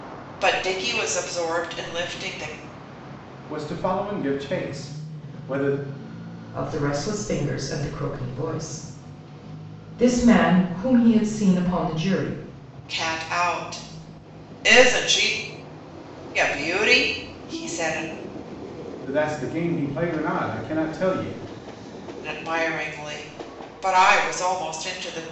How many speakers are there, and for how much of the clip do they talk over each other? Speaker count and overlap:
3, no overlap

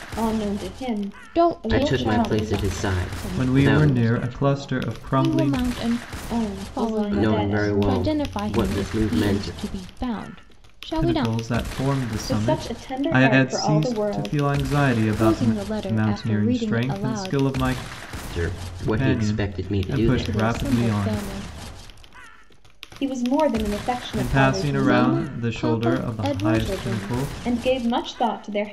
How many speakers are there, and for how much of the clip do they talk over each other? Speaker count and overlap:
4, about 62%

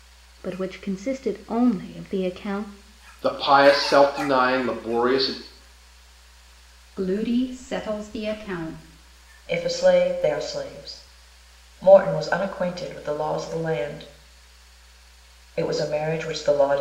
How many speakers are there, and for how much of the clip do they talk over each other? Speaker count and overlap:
4, no overlap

